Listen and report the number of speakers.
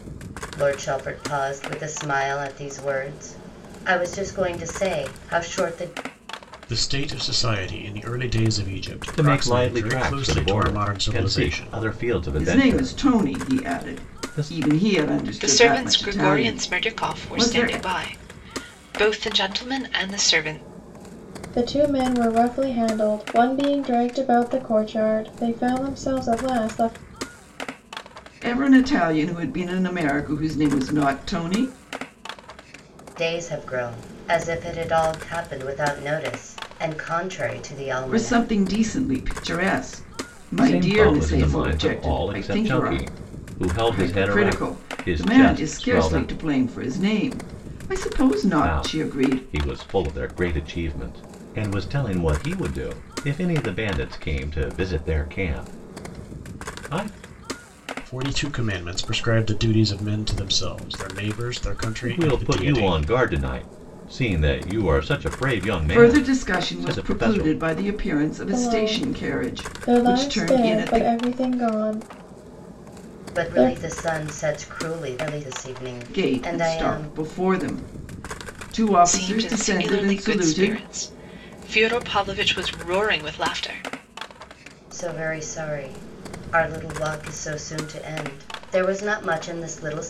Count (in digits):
6